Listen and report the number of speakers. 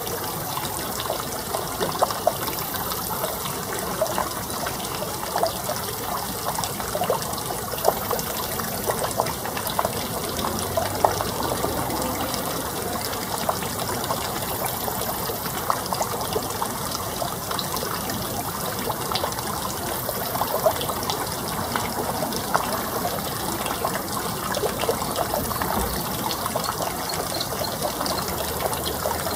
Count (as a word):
zero